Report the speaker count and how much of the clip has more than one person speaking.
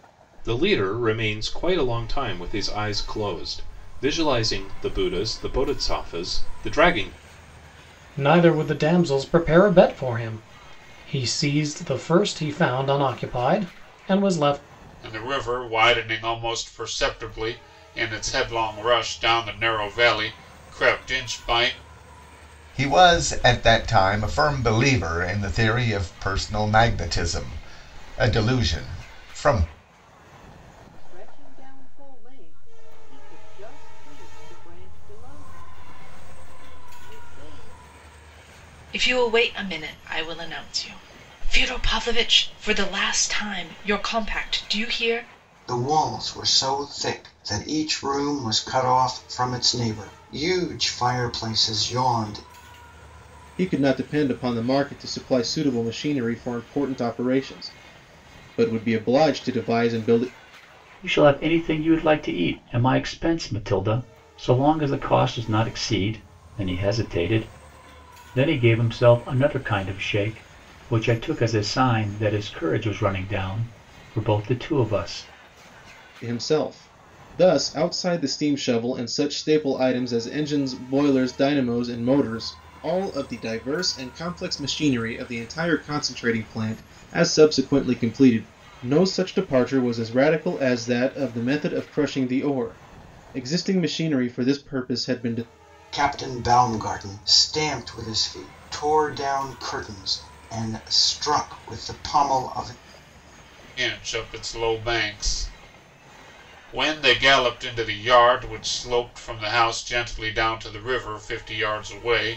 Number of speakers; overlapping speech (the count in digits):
9, no overlap